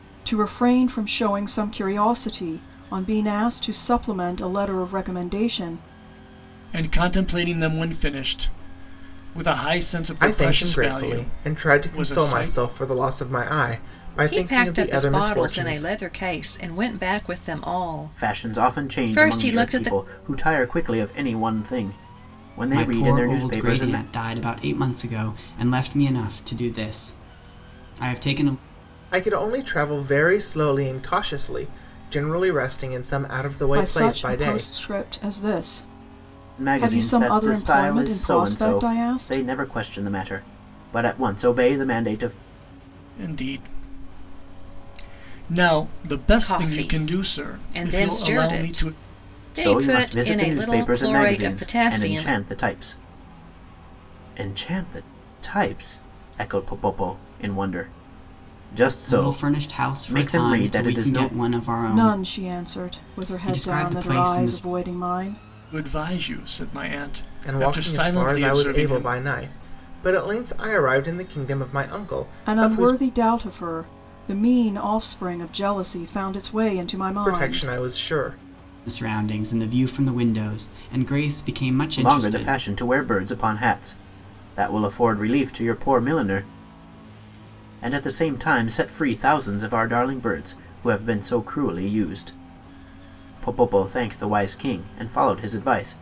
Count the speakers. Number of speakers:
6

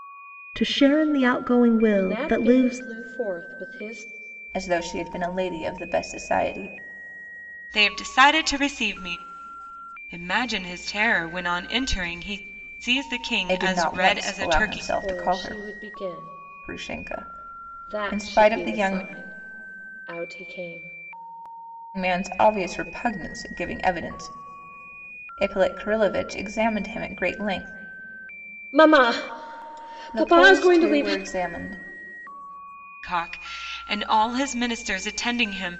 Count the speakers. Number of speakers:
4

